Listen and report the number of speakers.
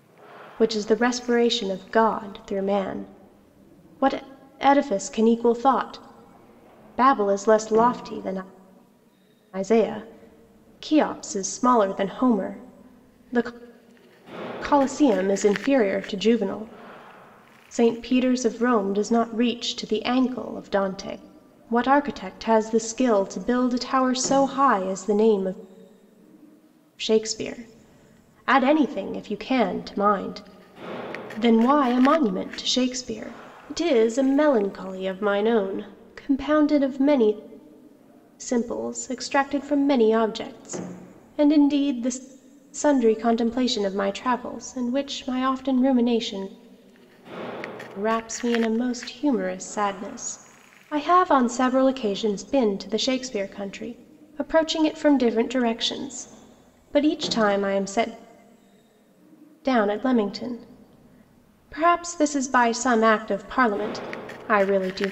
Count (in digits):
1